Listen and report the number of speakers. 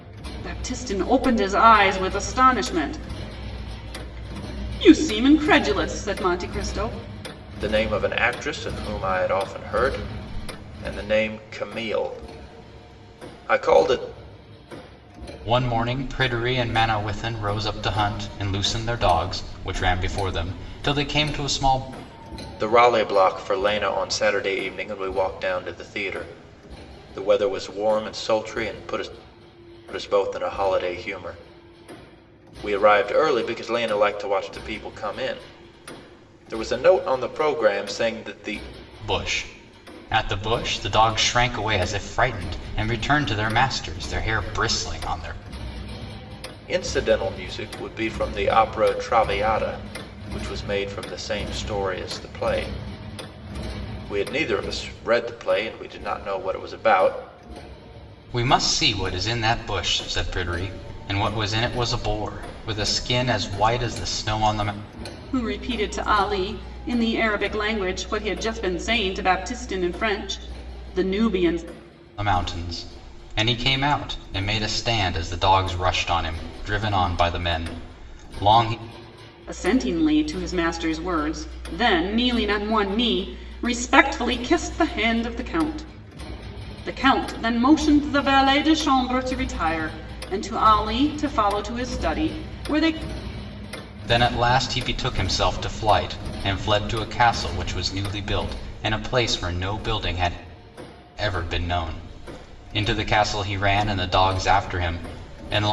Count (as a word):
three